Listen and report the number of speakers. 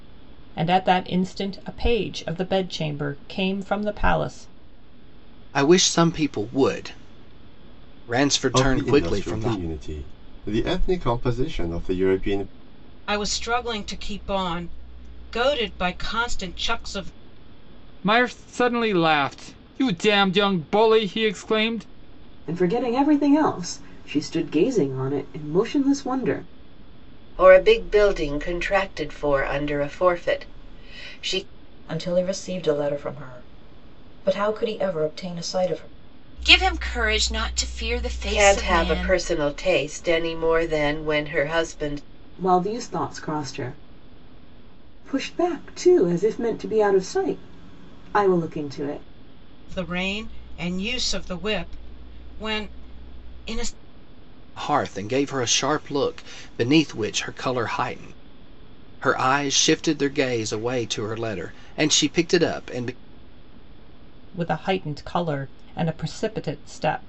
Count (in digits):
9